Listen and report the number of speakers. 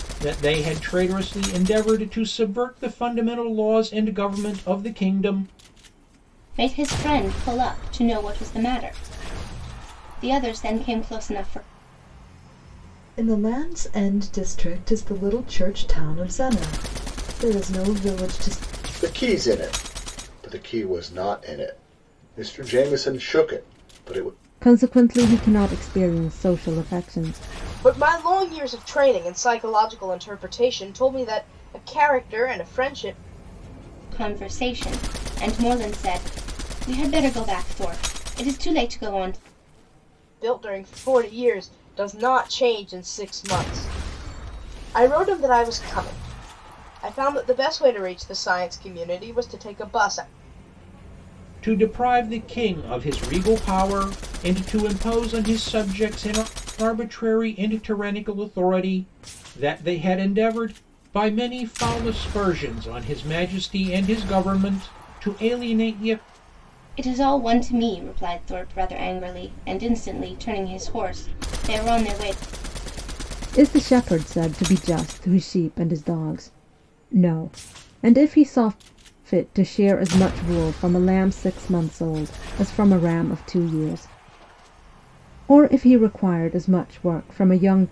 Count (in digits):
6